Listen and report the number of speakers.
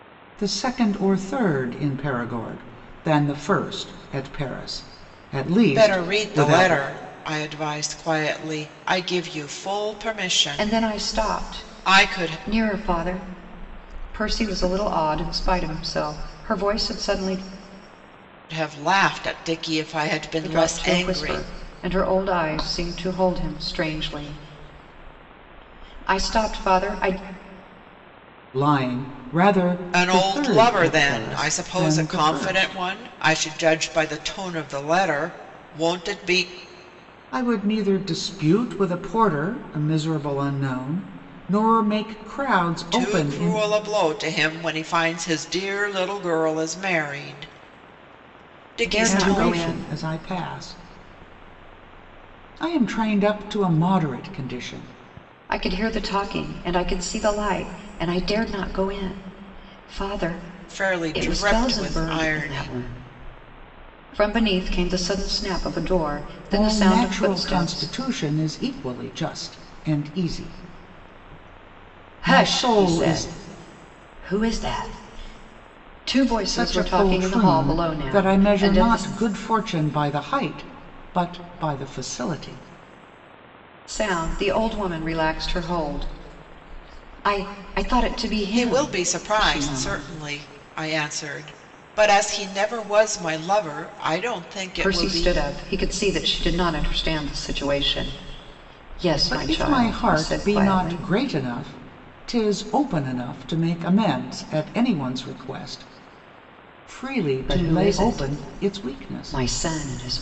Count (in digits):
3